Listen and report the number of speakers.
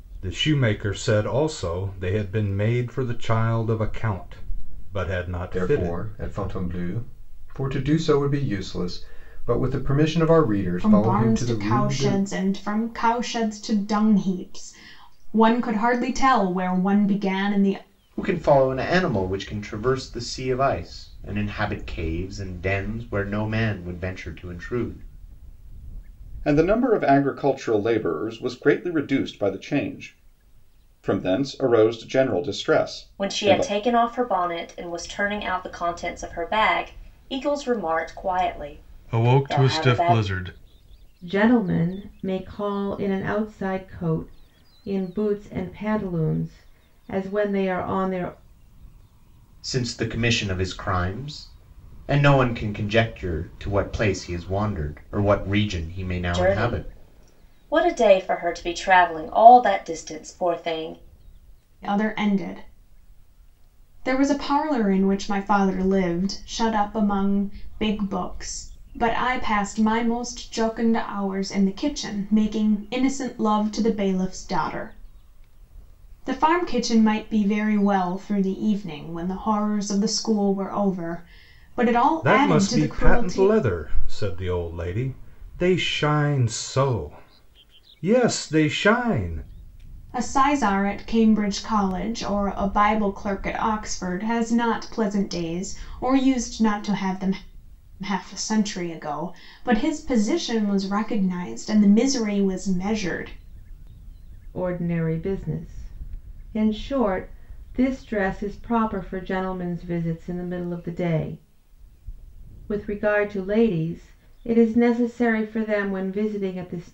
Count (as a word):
eight